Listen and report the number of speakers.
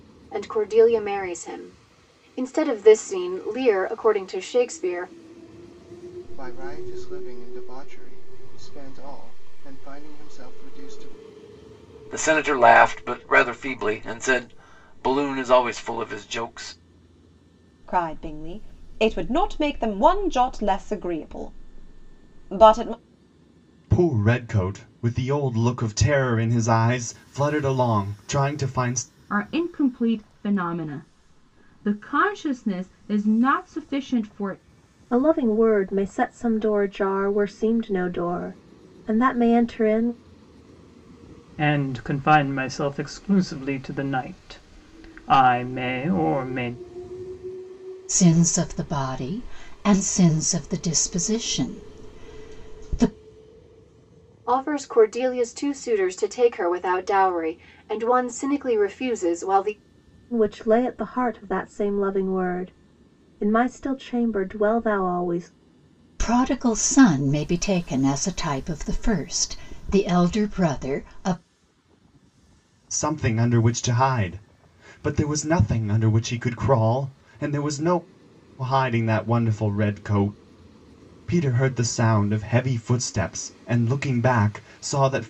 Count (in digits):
9